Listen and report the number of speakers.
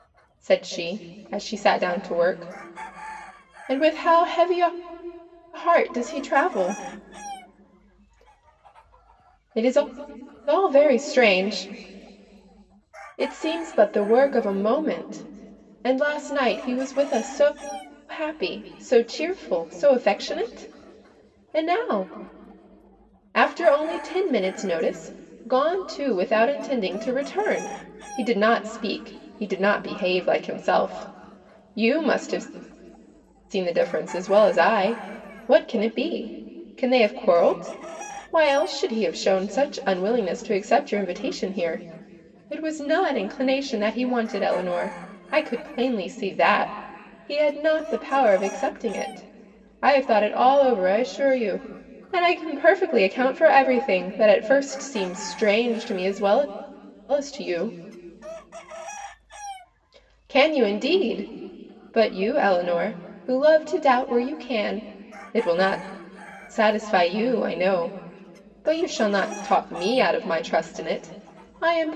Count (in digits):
1